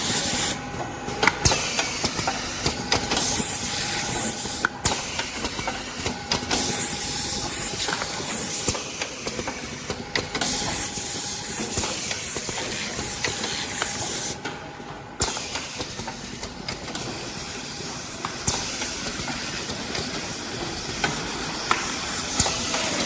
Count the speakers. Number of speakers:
zero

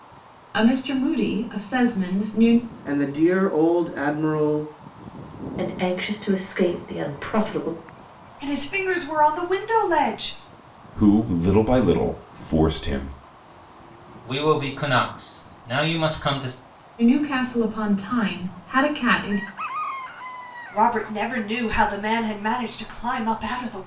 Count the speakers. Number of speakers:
six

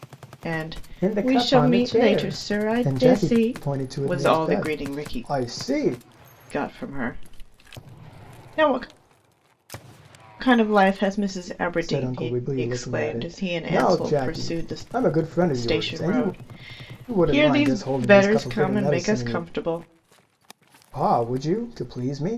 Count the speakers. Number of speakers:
two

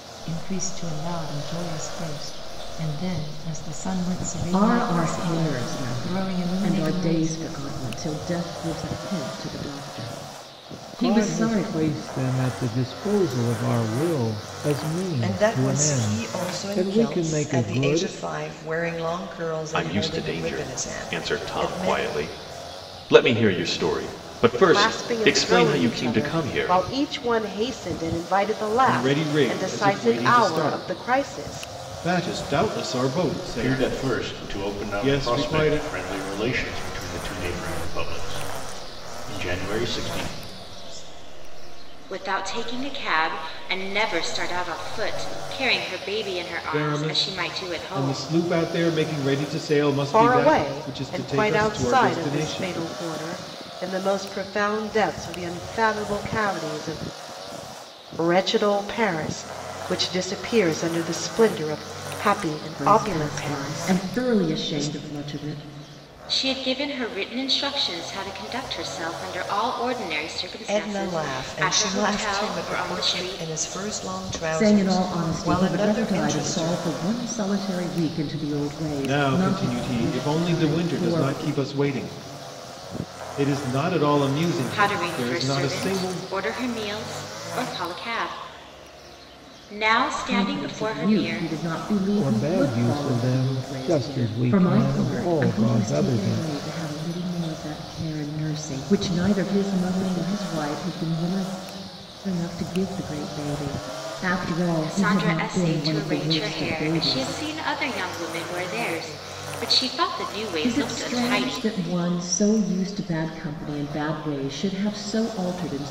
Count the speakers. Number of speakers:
ten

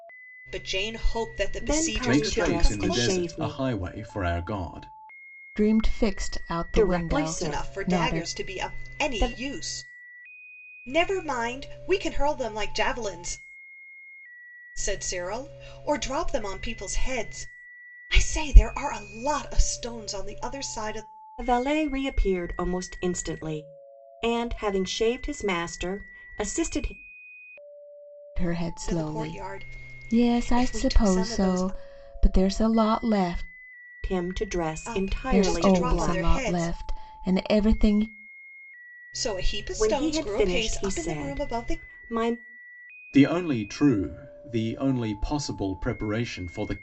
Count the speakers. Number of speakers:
four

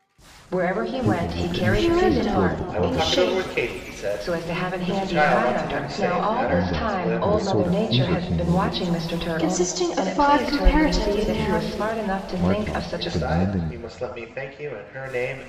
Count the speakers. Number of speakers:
four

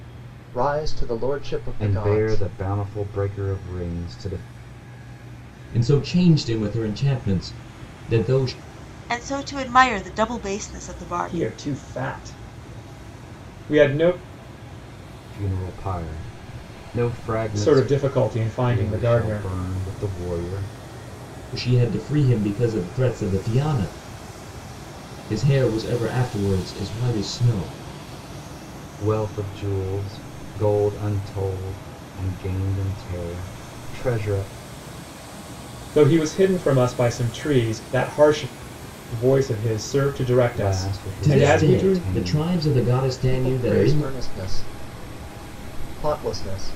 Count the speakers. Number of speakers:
five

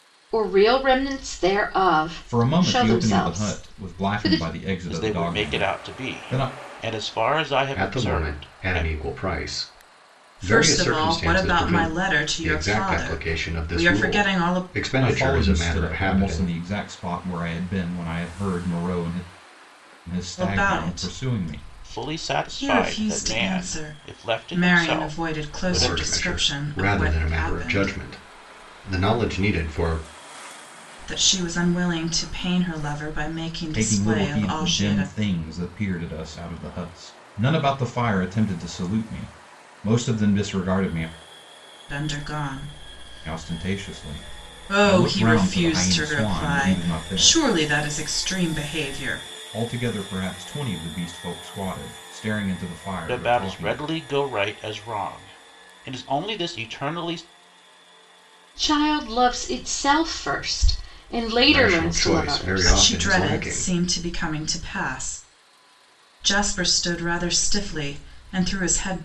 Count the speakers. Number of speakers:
five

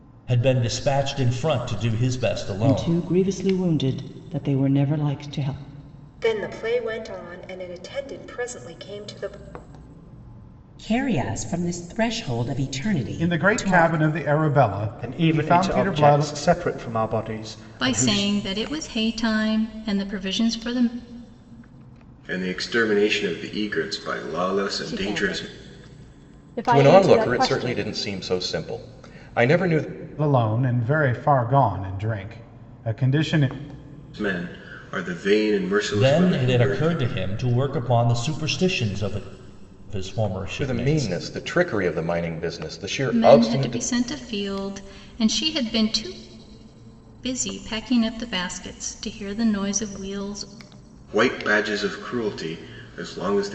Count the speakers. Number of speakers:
ten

